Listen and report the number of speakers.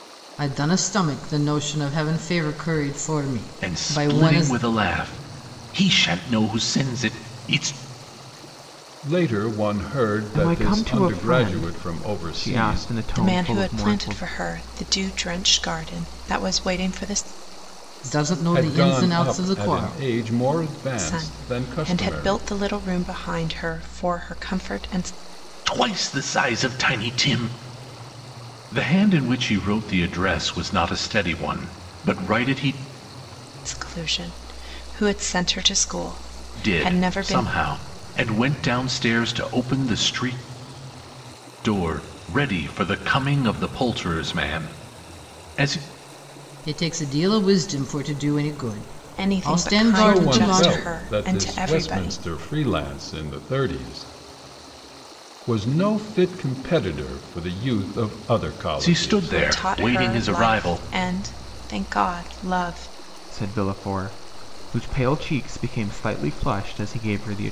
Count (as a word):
five